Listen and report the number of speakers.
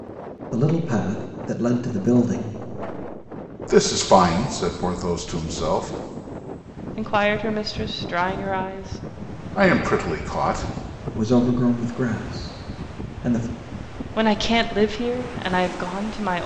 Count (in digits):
3